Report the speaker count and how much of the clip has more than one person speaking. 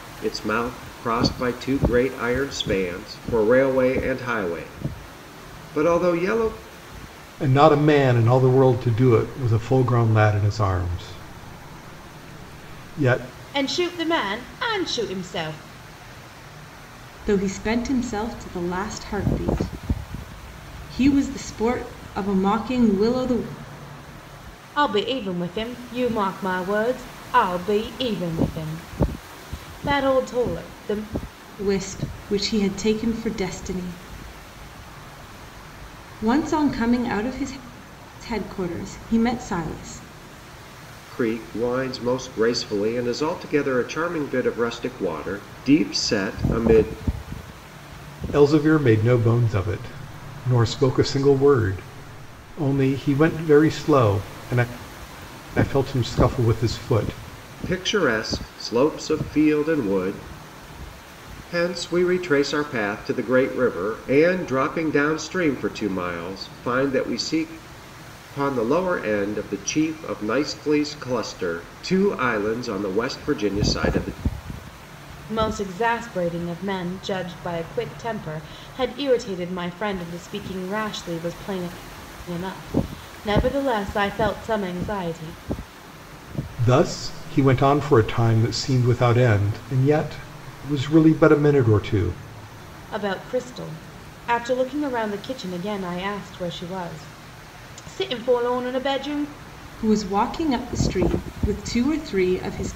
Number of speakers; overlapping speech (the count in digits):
4, no overlap